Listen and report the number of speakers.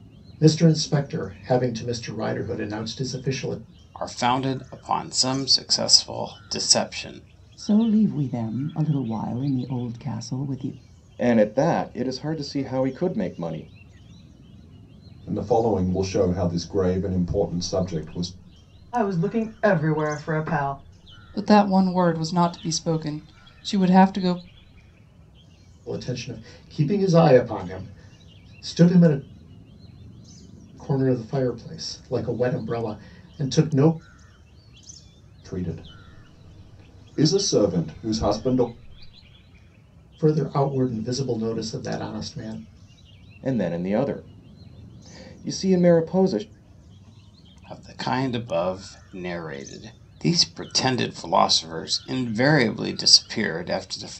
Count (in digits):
7